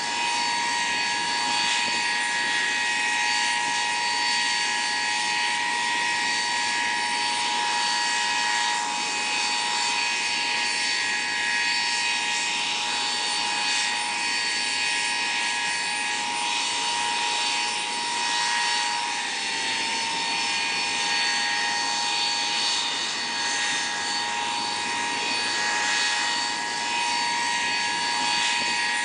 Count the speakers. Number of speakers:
zero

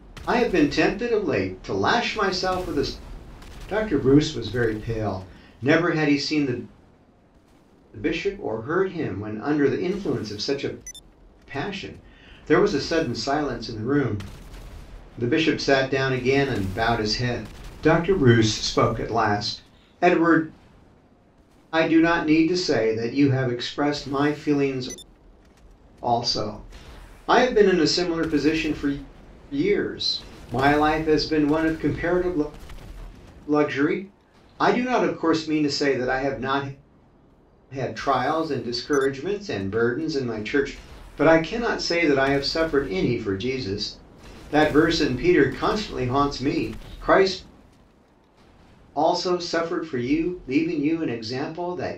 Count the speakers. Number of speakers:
one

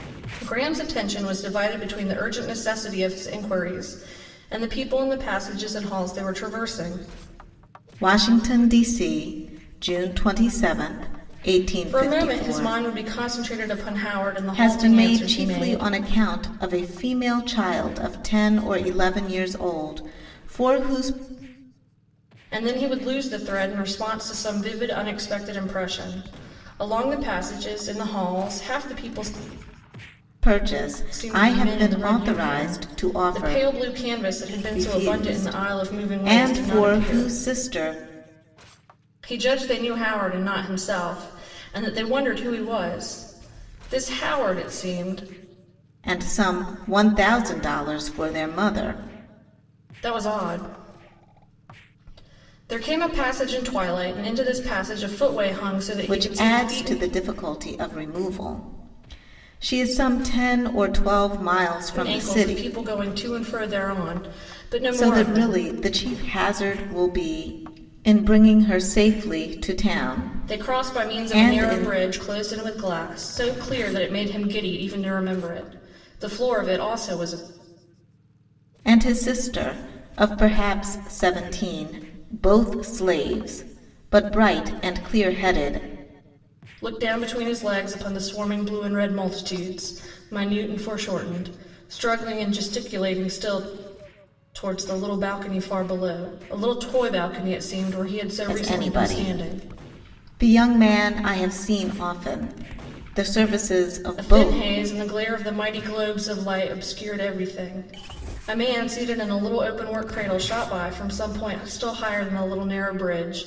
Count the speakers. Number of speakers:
two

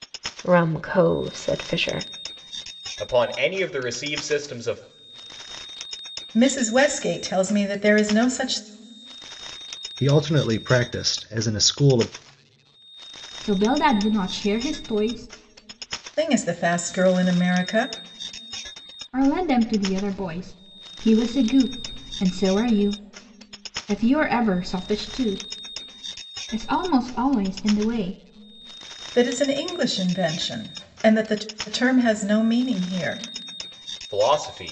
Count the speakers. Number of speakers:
five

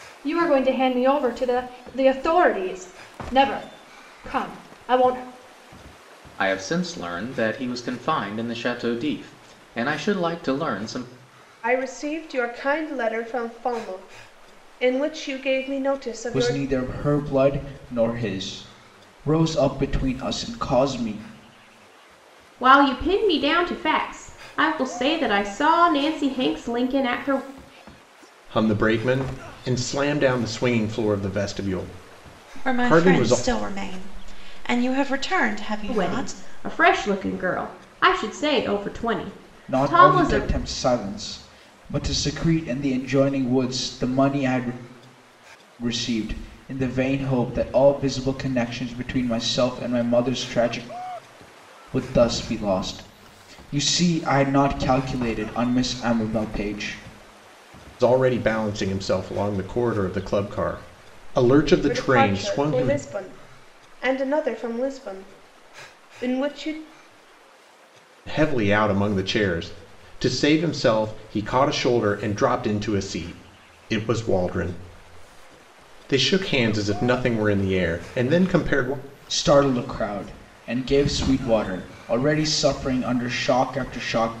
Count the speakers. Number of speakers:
seven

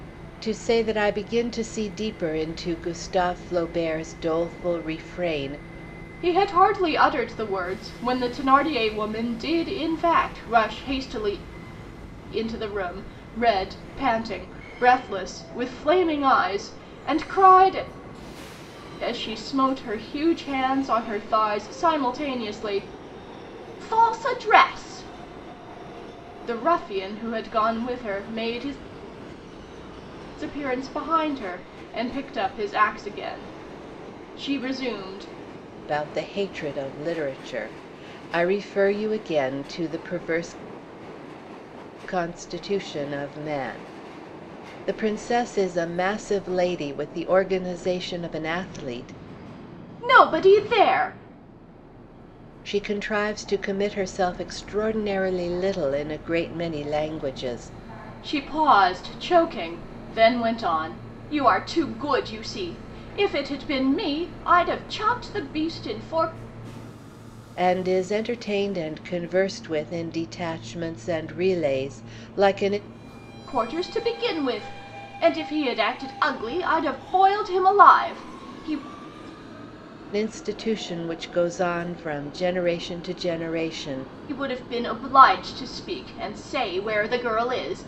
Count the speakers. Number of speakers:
two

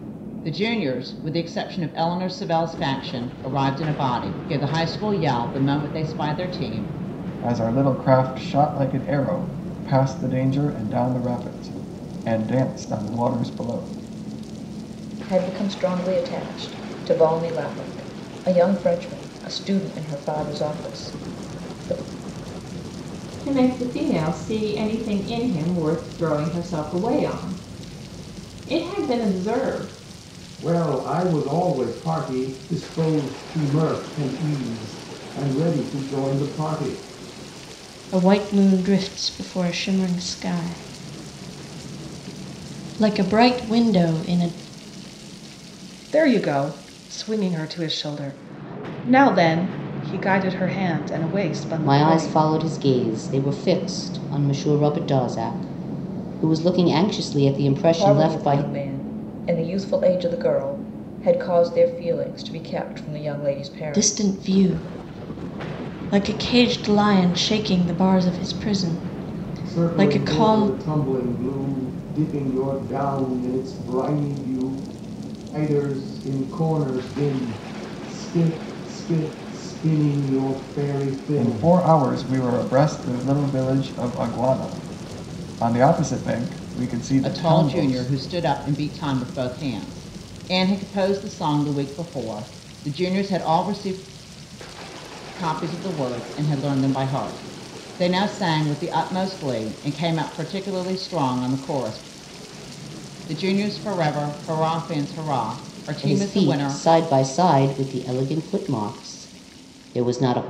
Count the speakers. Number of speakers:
eight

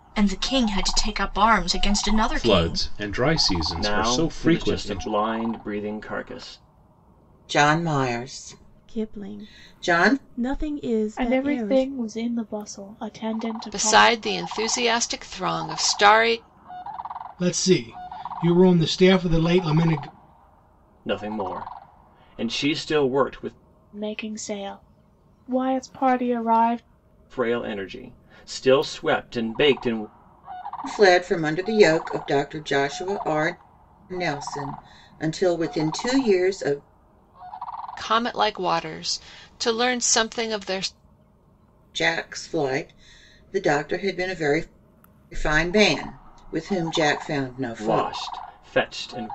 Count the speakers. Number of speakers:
eight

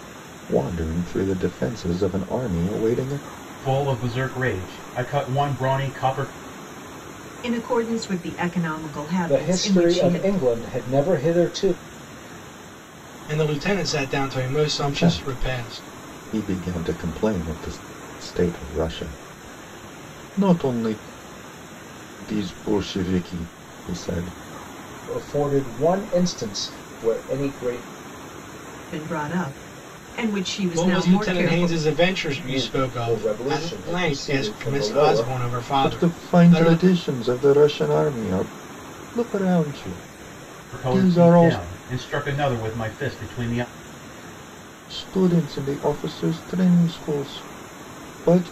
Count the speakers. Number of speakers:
five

